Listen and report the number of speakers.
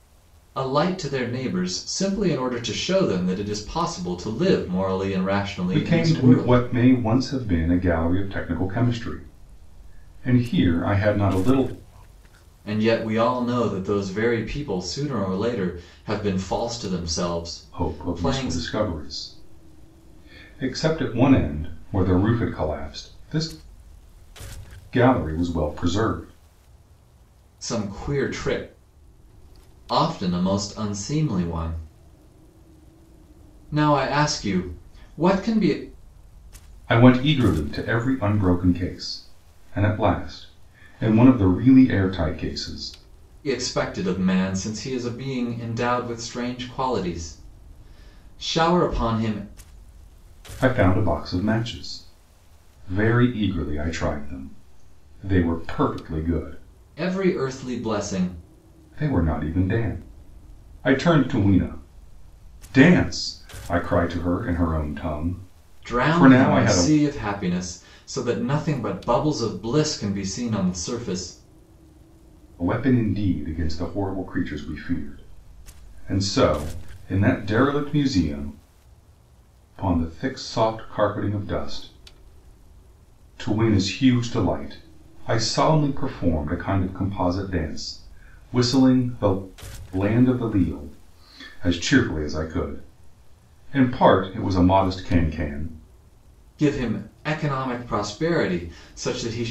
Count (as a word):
two